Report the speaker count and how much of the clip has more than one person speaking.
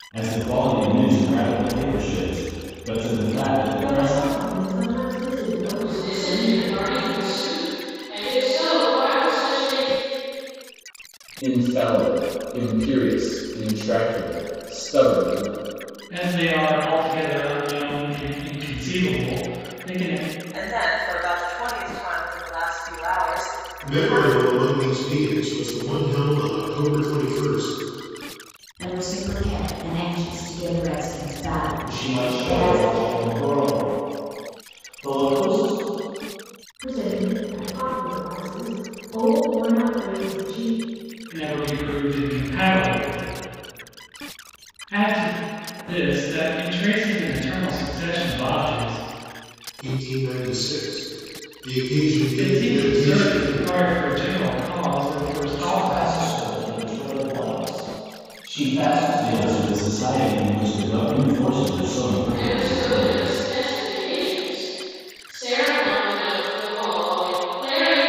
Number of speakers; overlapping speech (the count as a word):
nine, about 10%